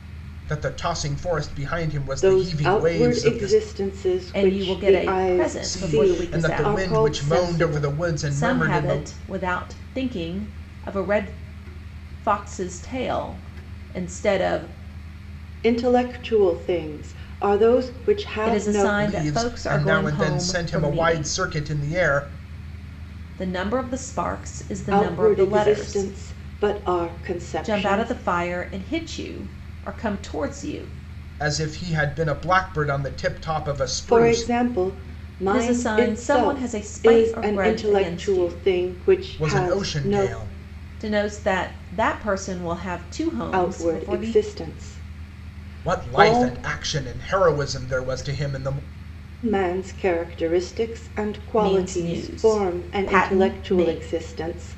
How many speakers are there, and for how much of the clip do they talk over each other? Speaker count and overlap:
3, about 35%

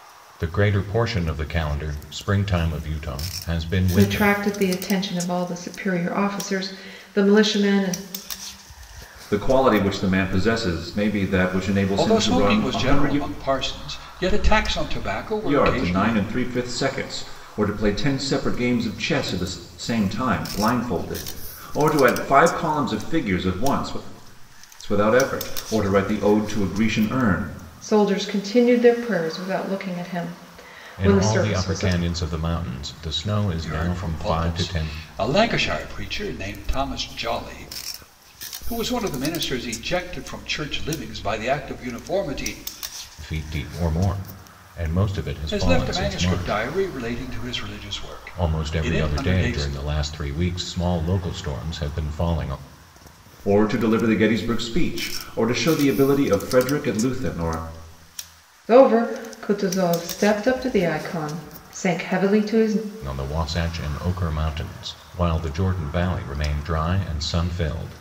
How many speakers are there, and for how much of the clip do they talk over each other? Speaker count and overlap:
4, about 11%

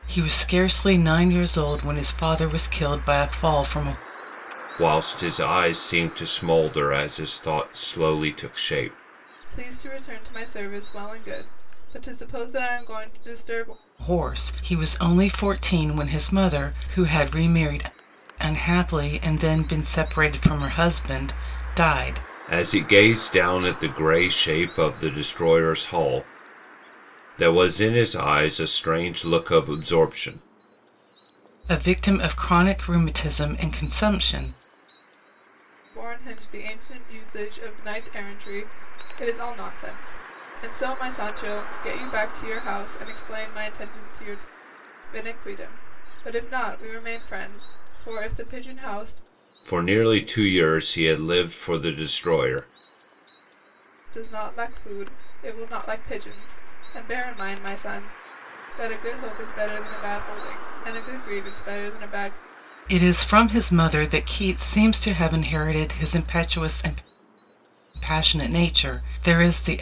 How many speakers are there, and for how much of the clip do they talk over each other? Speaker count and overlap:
3, no overlap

